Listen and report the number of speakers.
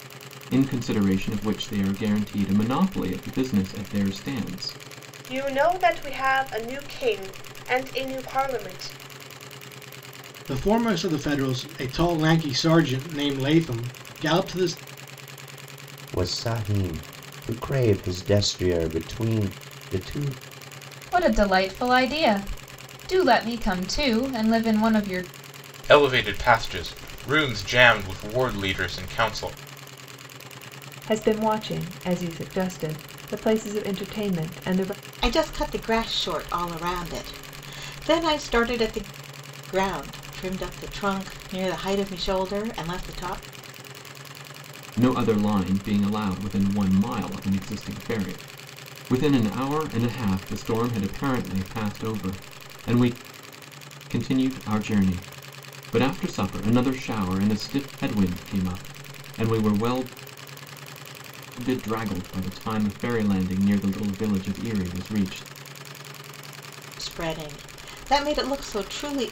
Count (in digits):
8